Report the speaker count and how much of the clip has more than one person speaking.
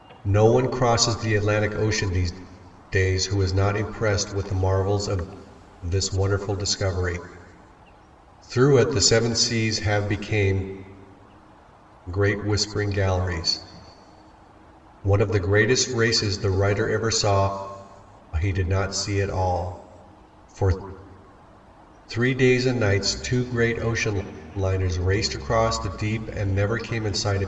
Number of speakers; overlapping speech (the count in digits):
1, no overlap